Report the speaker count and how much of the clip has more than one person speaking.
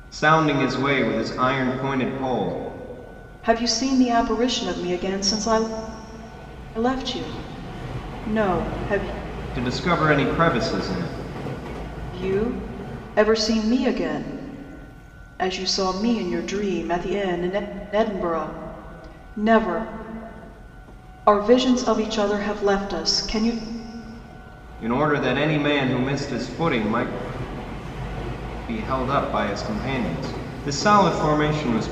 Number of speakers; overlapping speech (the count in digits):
2, no overlap